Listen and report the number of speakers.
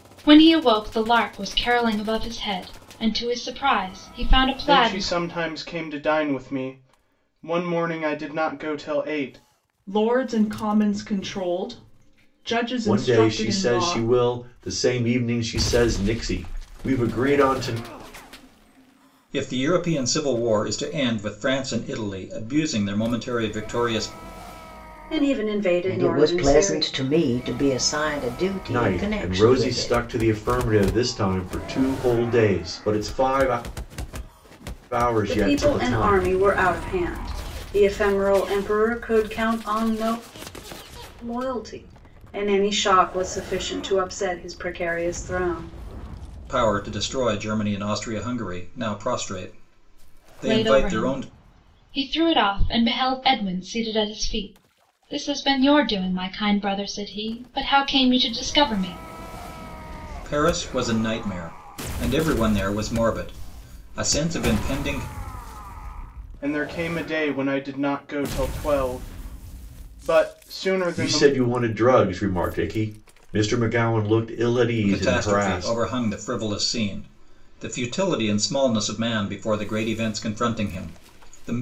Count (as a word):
seven